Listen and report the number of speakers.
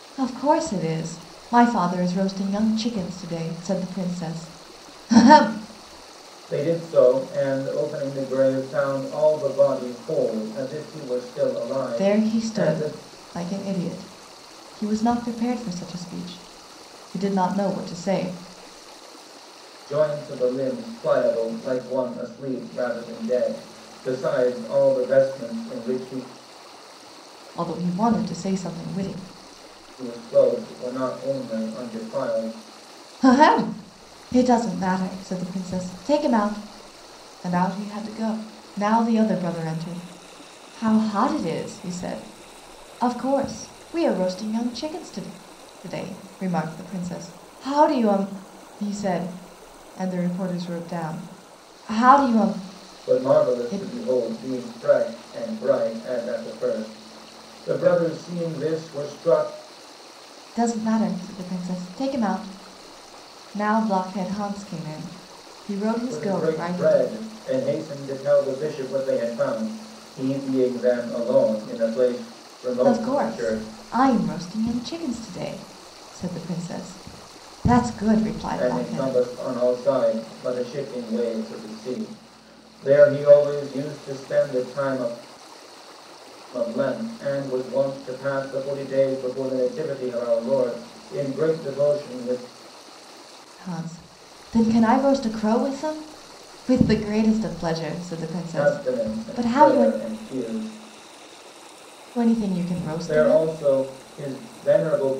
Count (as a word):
two